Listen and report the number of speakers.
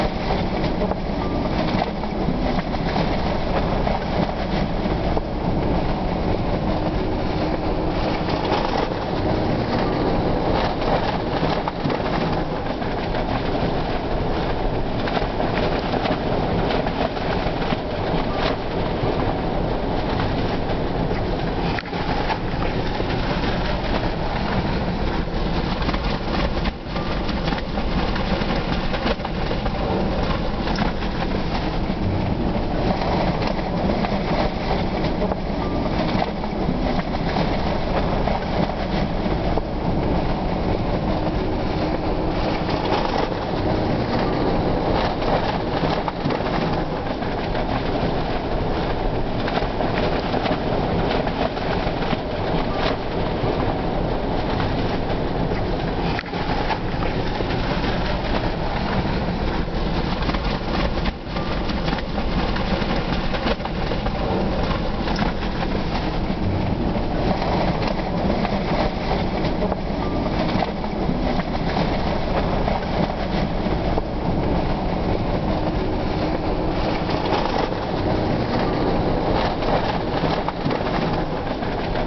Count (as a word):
zero